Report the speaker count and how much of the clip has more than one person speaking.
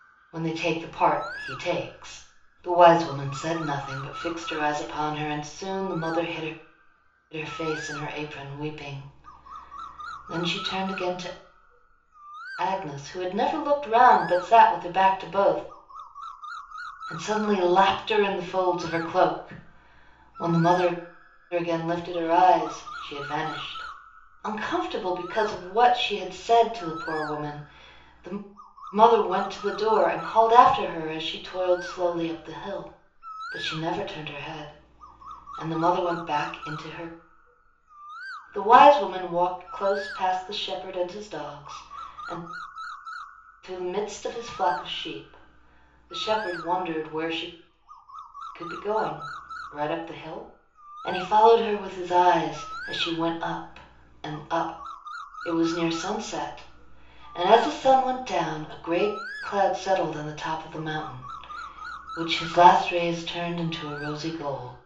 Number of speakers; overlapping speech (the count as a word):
one, no overlap